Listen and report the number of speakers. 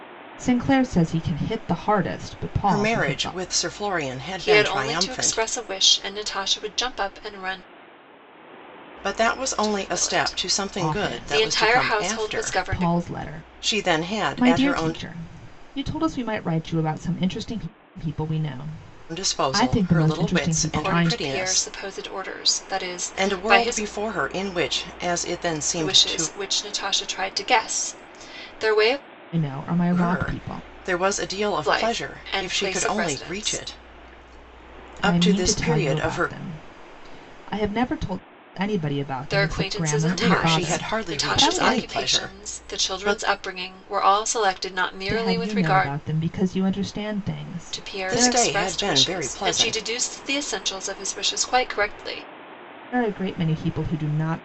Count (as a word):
three